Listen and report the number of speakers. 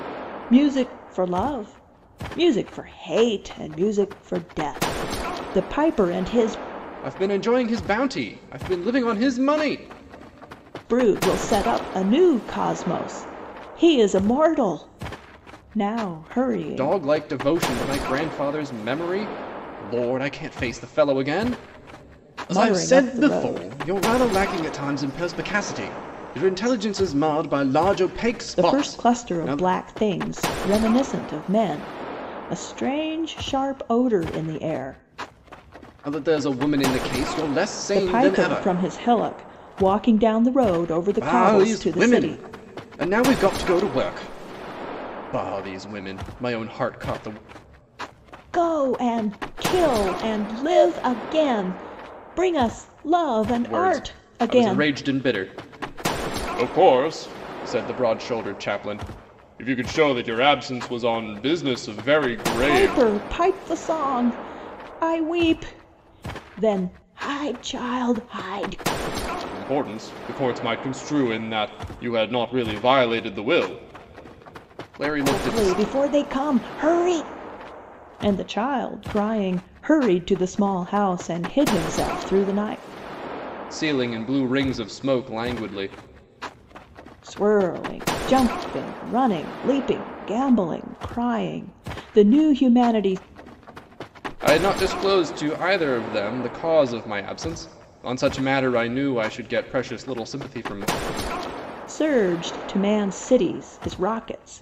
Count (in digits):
2